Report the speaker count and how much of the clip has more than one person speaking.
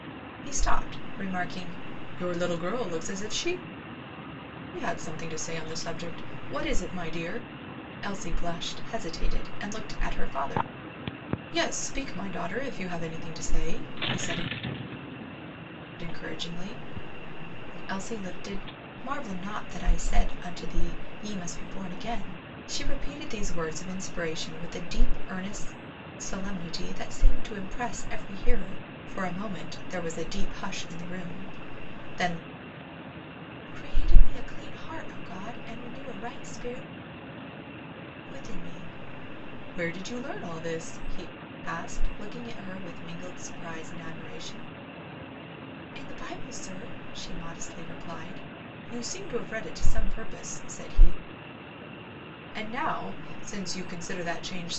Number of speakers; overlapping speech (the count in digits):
1, no overlap